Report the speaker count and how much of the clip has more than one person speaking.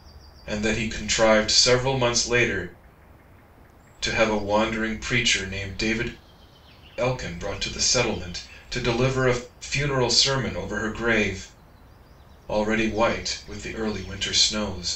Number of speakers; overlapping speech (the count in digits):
1, no overlap